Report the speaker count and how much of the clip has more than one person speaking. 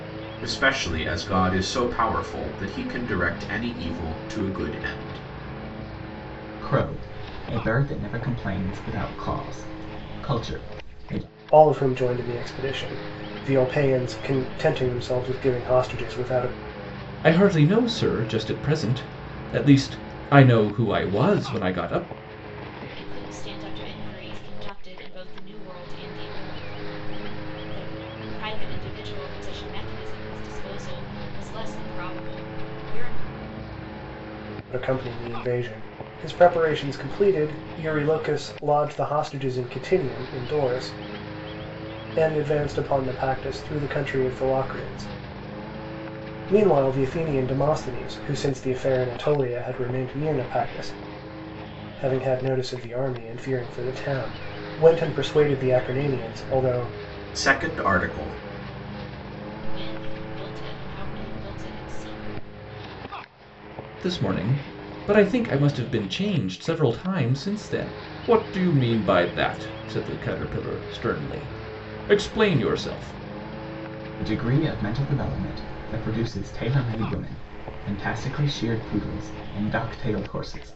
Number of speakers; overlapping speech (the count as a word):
five, no overlap